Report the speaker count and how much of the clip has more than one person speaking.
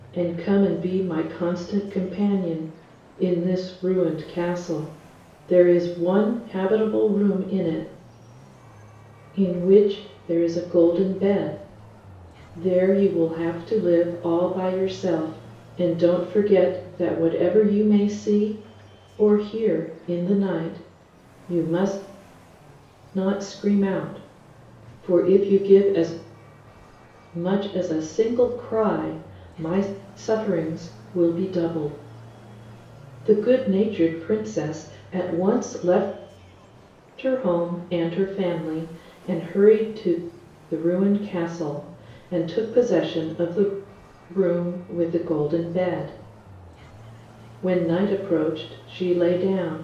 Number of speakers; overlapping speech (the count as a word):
one, no overlap